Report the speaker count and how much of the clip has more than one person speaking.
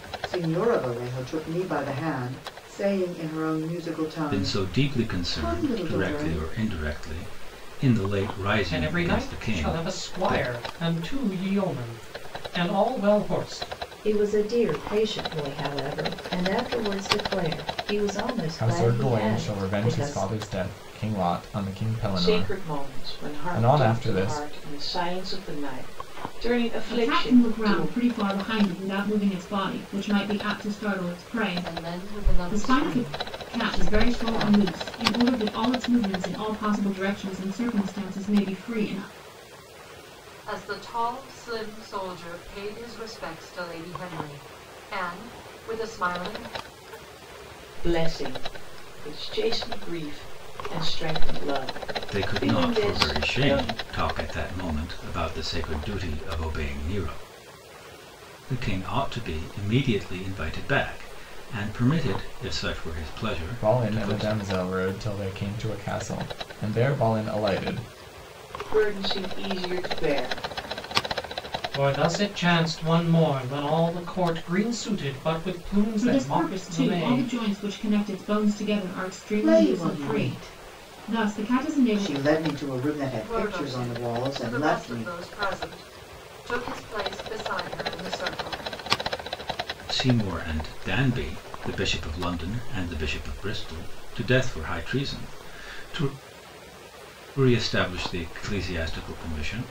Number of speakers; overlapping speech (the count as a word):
eight, about 21%